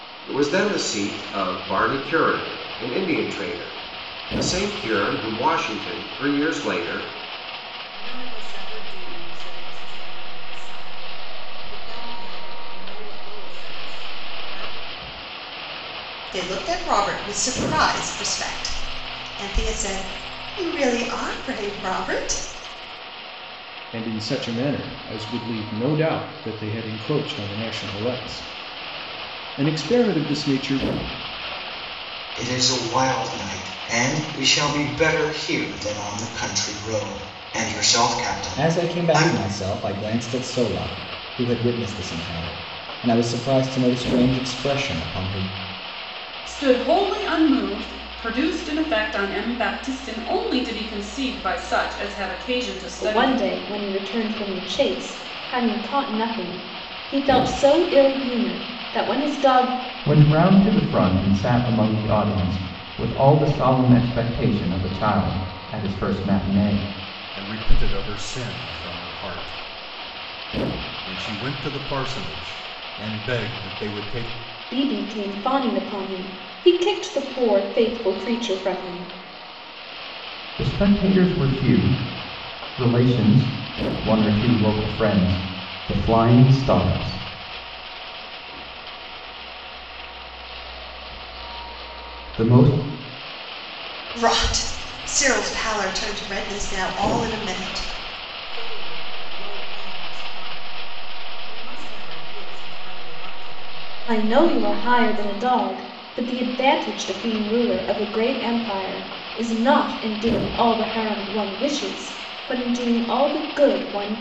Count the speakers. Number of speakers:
10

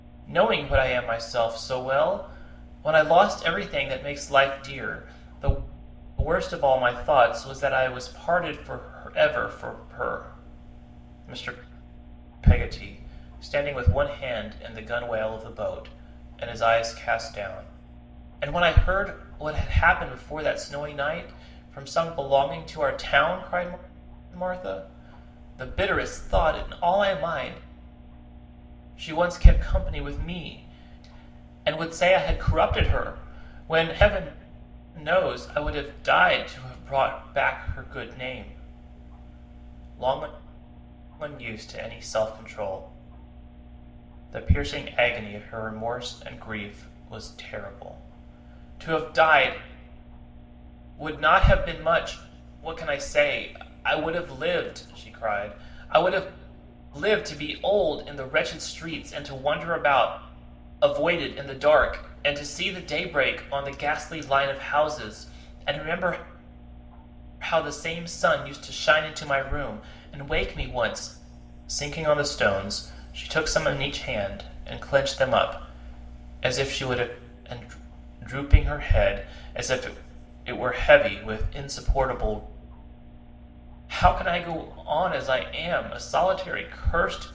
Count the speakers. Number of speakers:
1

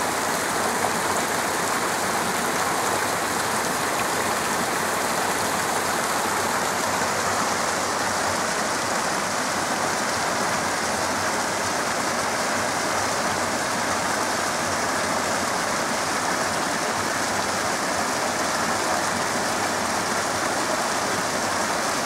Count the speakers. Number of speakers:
0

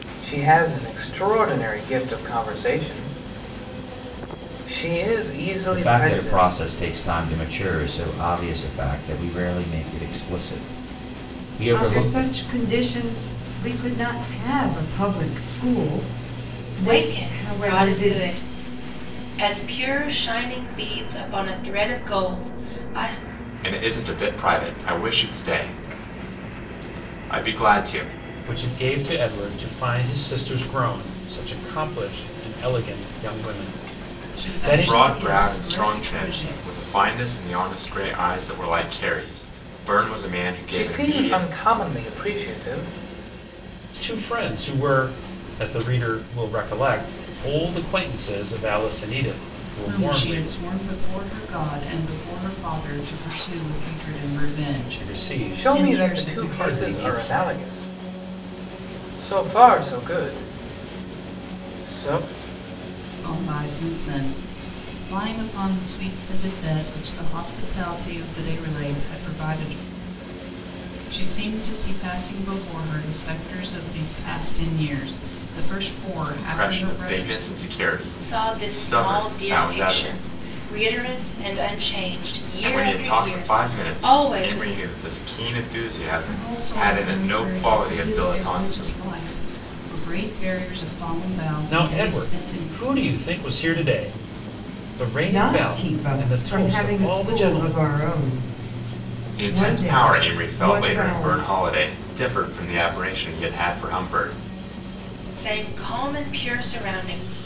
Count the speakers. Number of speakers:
7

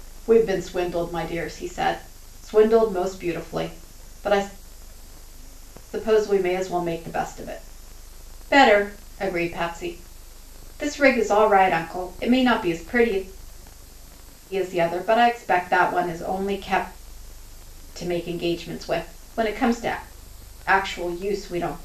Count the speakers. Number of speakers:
1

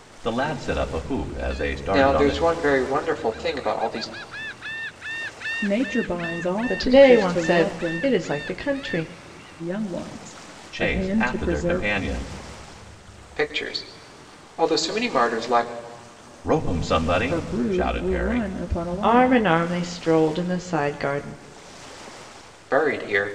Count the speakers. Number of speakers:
4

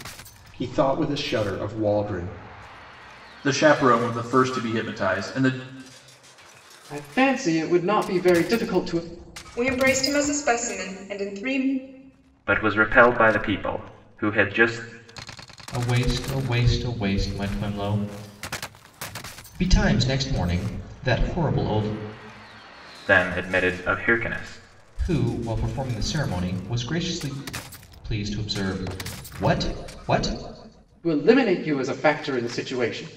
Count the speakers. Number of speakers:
6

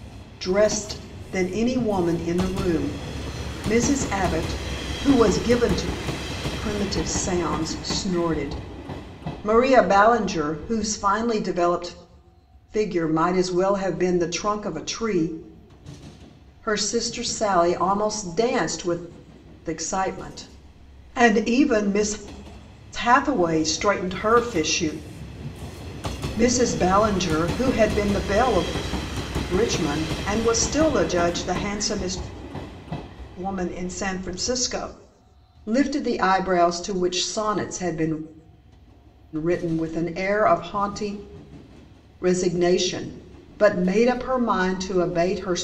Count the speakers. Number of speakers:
1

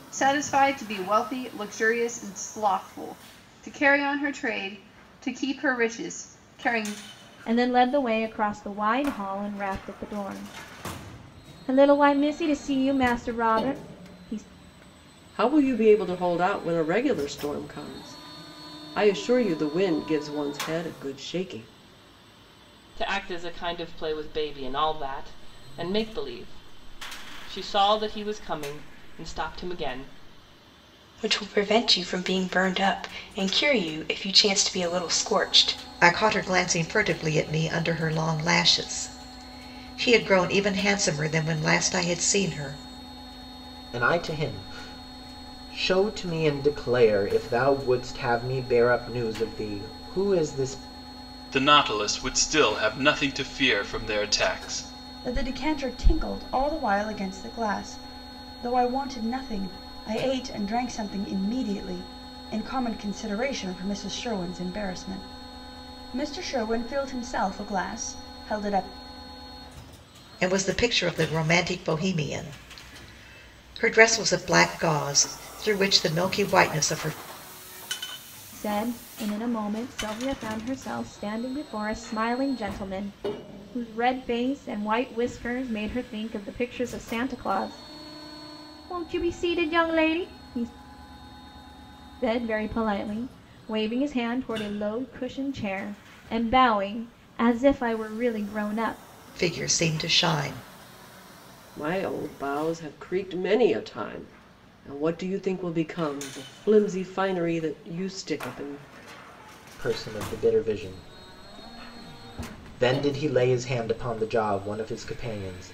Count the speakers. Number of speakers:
9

